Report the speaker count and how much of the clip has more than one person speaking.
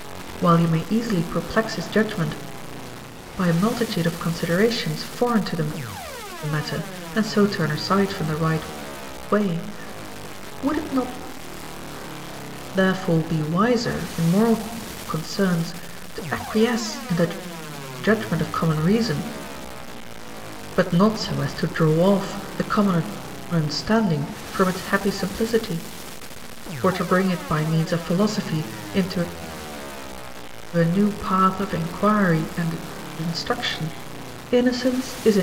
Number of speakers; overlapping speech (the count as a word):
one, no overlap